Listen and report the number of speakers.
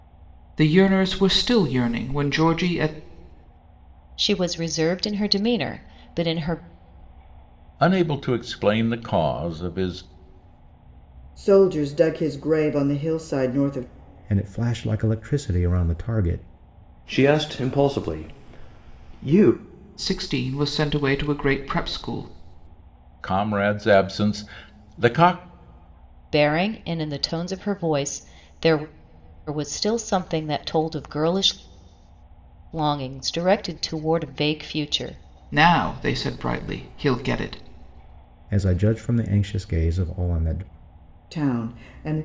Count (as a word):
six